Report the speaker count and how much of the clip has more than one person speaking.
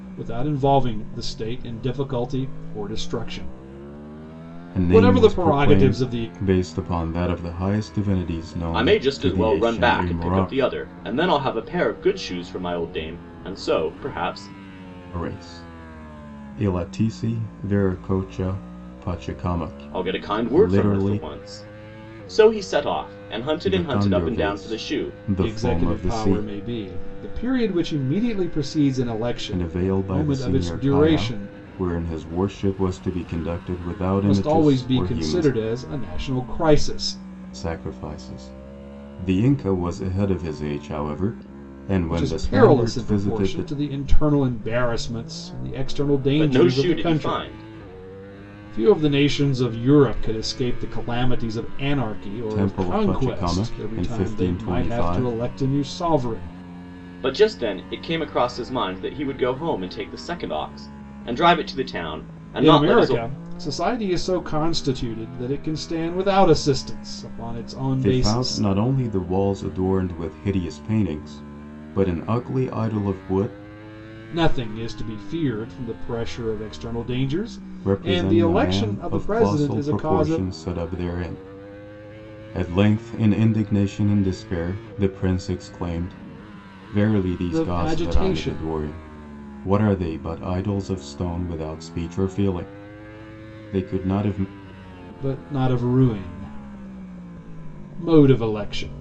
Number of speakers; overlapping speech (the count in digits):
3, about 22%